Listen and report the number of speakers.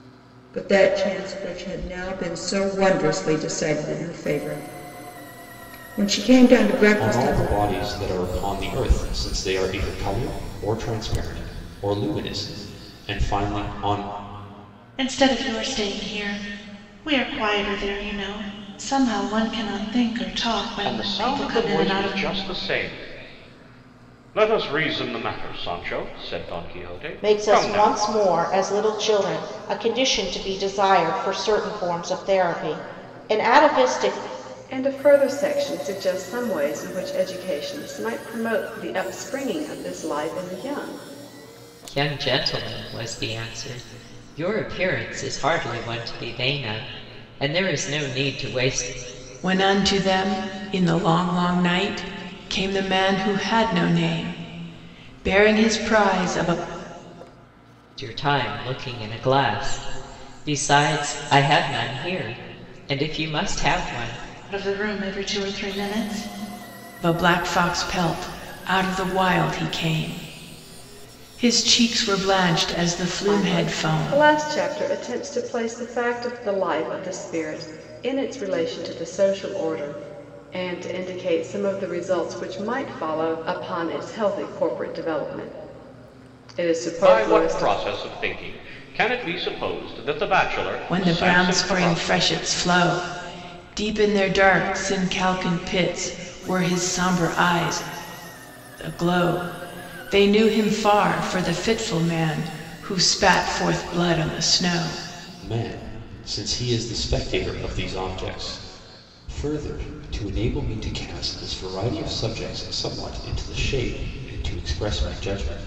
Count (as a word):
eight